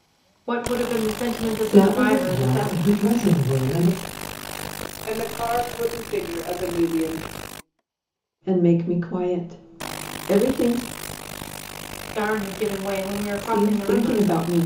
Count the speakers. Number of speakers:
four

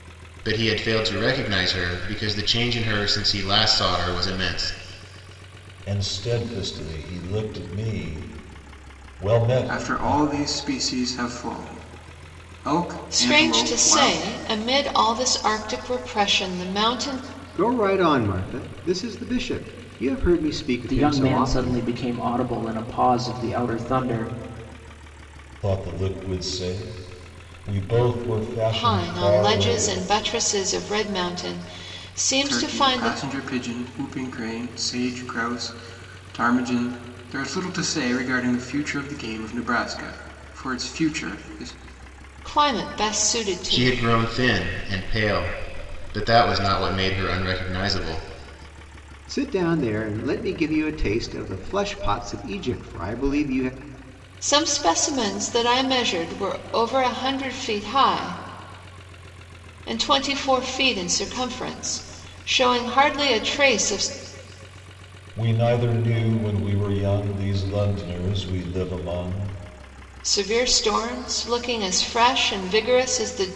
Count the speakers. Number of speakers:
six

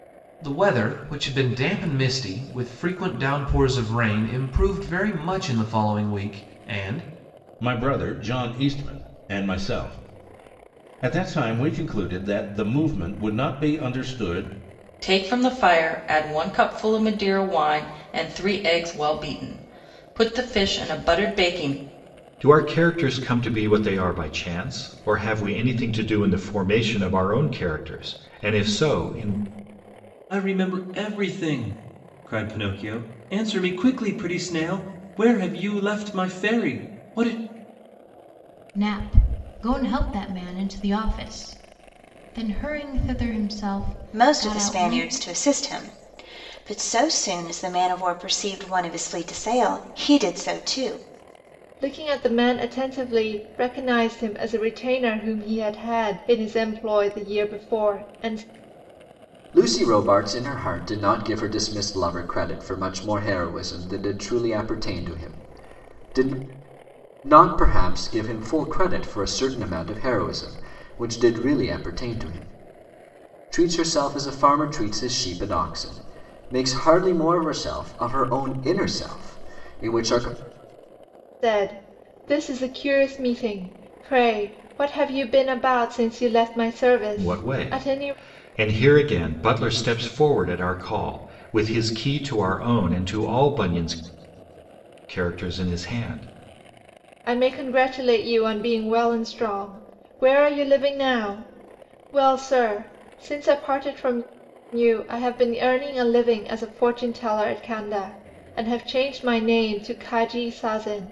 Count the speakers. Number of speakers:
nine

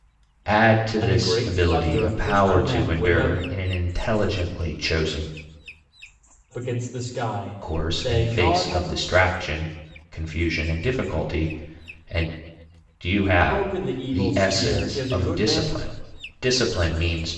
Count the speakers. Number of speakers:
two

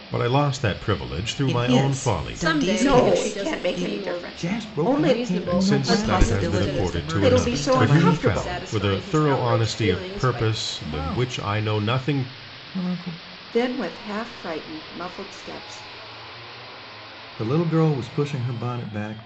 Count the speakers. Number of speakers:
five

